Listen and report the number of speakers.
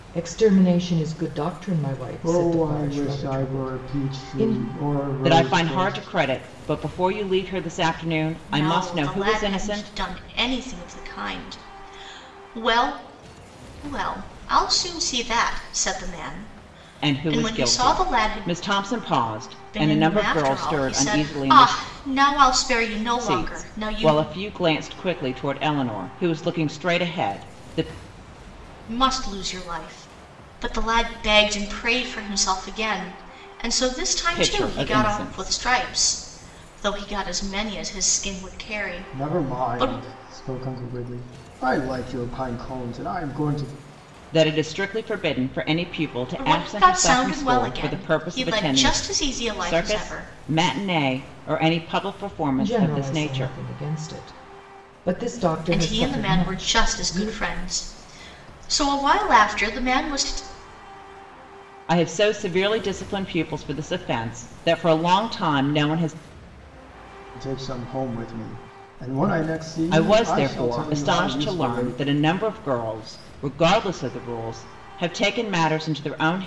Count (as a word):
four